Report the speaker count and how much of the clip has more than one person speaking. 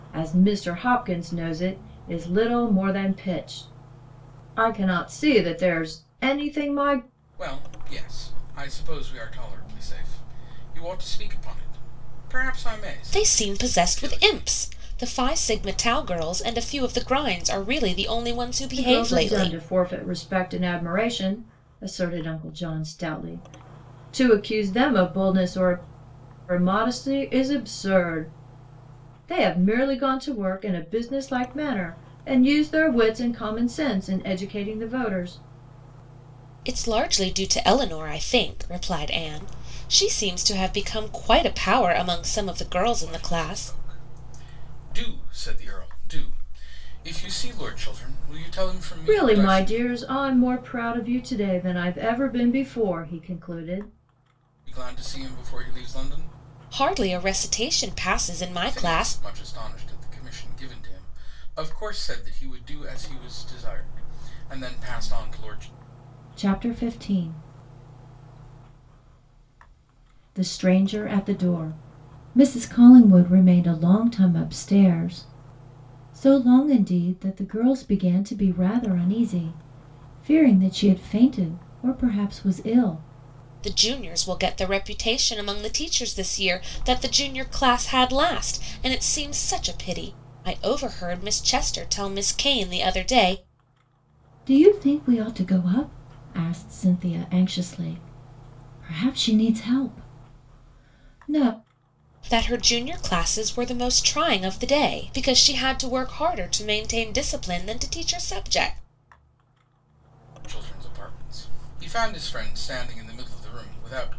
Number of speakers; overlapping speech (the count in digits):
3, about 4%